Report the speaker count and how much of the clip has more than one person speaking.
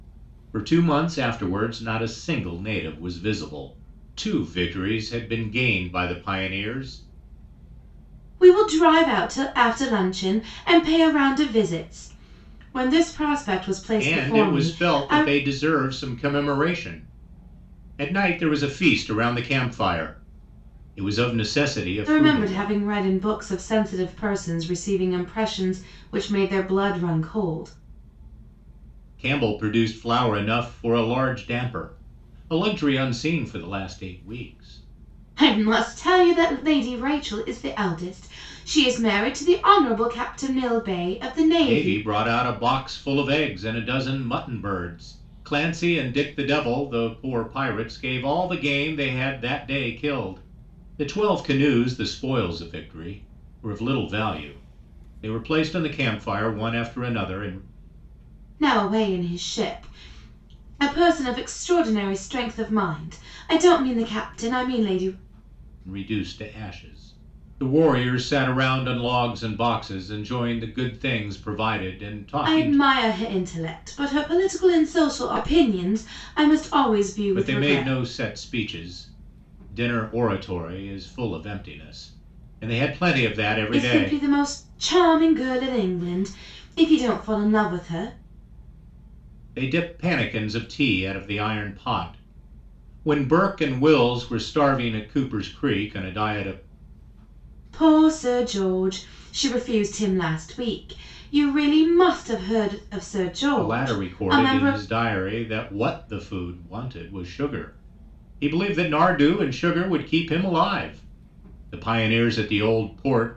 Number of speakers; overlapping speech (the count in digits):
2, about 5%